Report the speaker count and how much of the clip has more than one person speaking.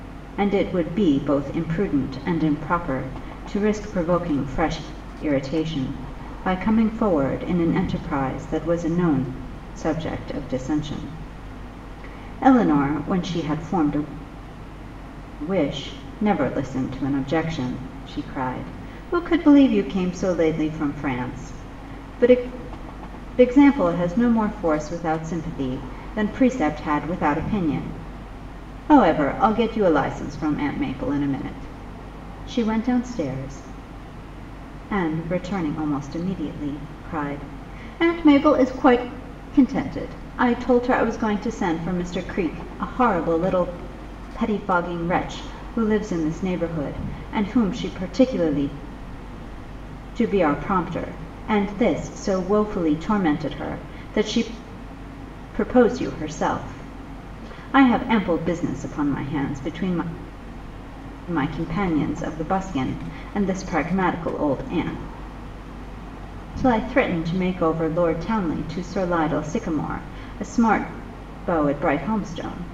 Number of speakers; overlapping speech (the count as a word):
one, no overlap